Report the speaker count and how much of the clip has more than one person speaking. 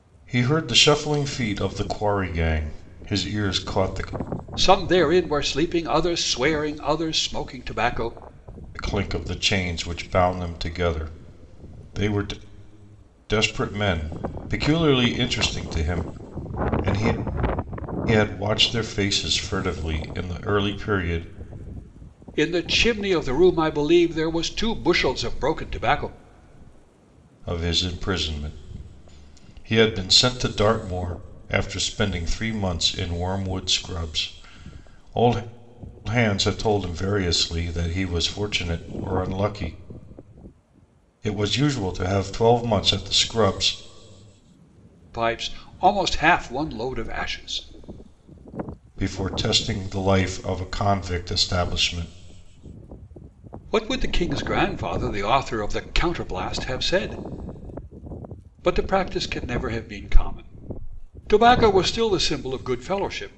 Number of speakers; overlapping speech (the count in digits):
2, no overlap